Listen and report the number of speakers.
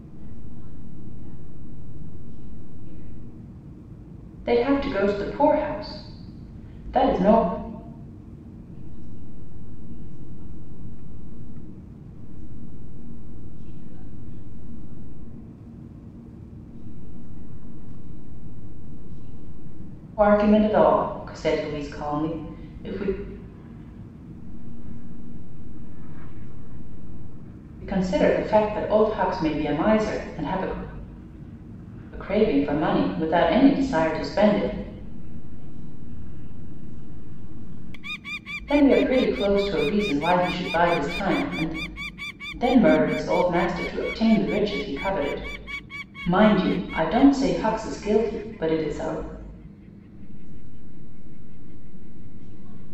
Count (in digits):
2